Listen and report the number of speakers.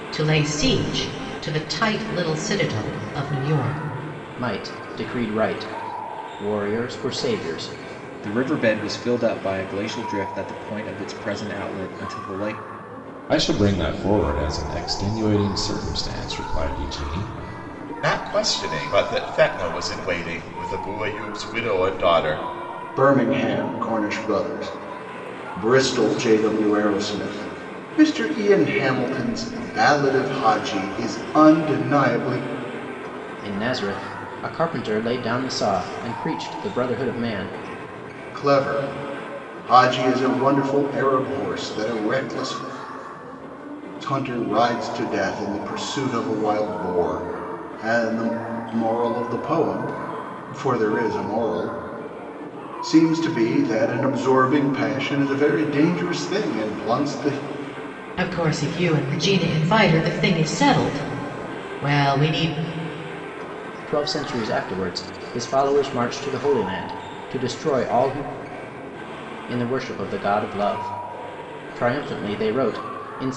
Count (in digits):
6